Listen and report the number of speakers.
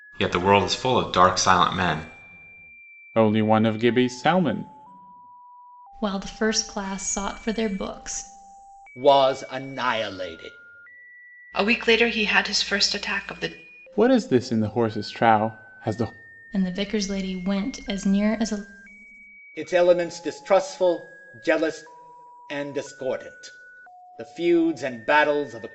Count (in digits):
5